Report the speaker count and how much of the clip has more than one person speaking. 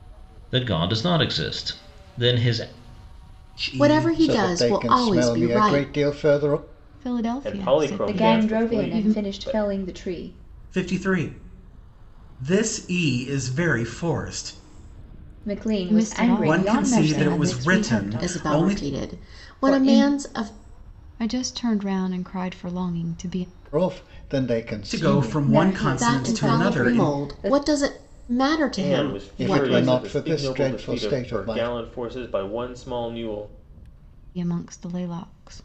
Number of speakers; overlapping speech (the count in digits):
7, about 40%